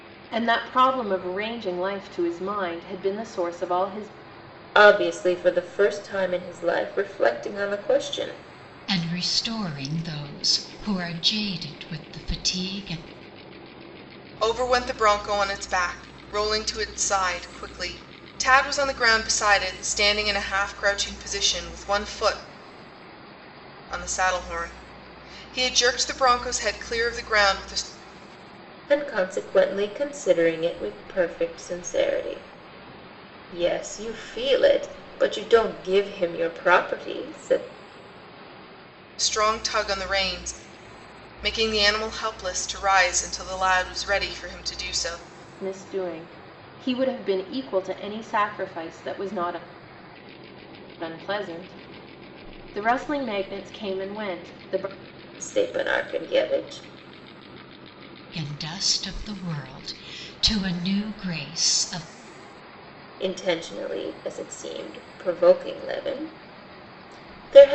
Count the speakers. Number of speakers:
4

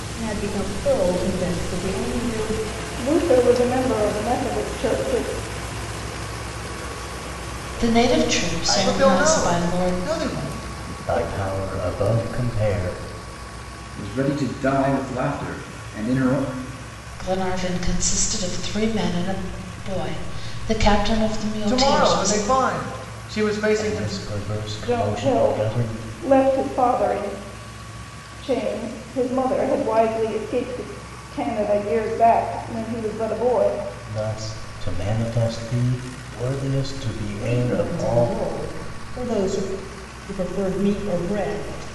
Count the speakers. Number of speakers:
7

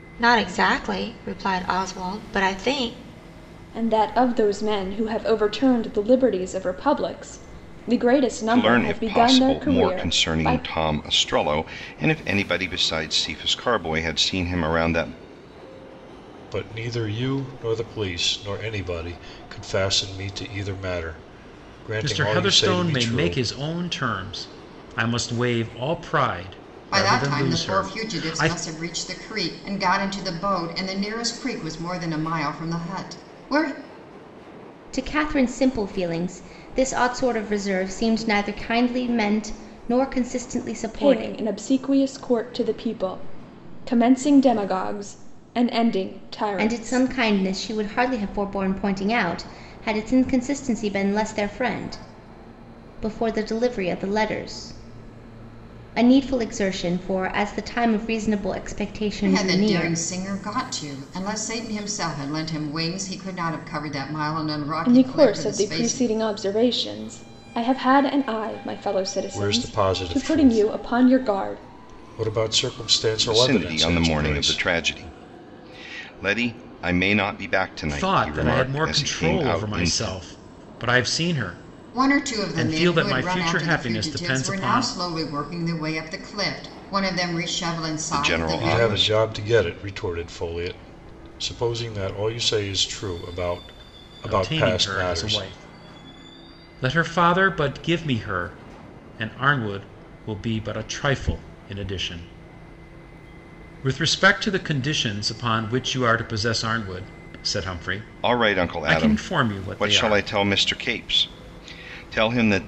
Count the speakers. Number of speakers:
7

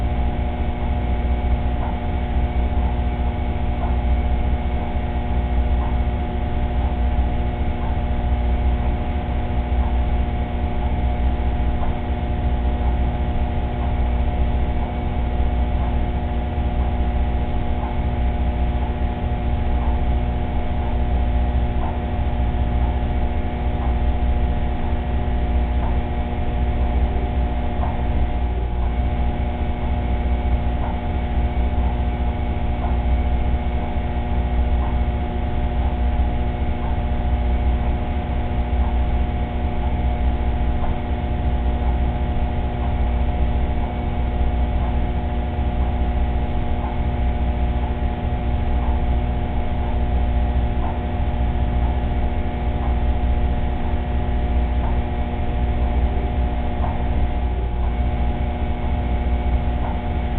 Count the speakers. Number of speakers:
0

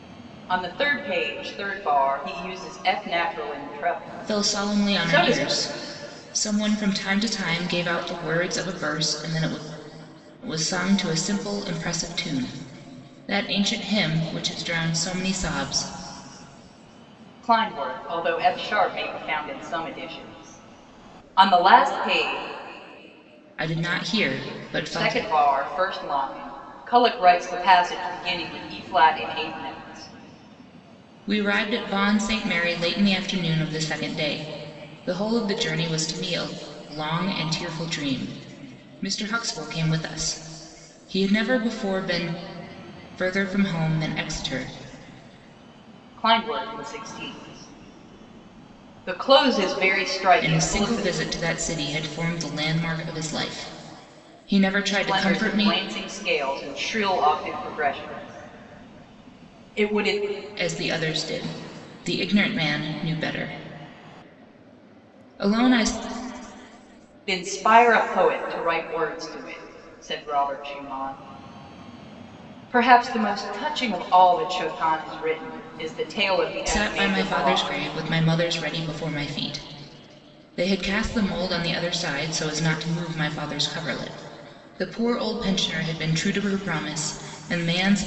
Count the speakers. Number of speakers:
2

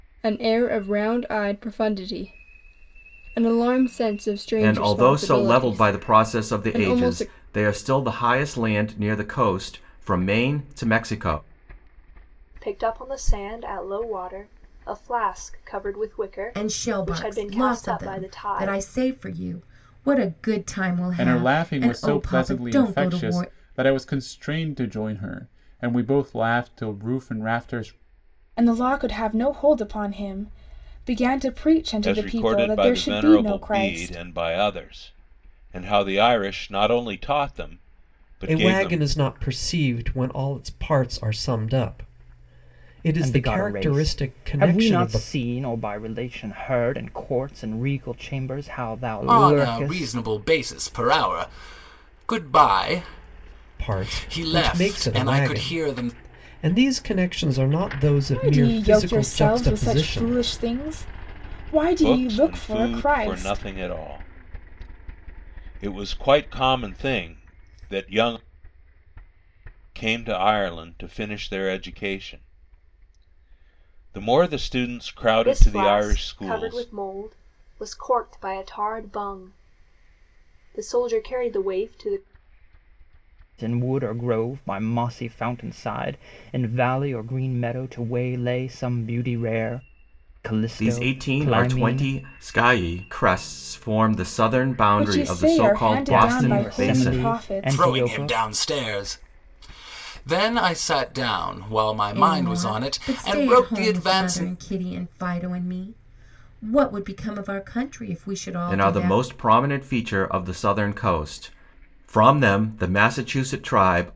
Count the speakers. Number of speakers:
10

